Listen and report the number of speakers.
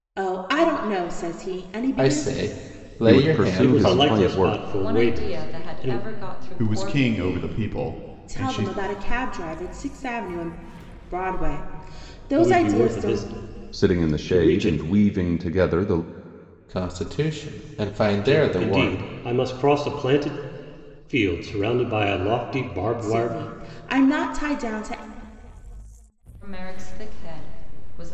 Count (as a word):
six